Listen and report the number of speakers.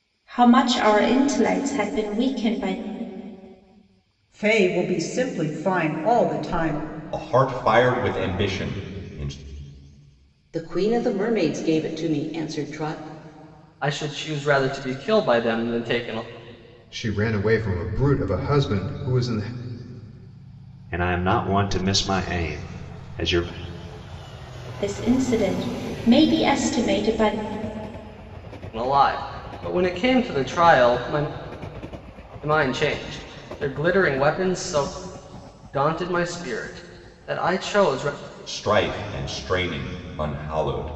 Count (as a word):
seven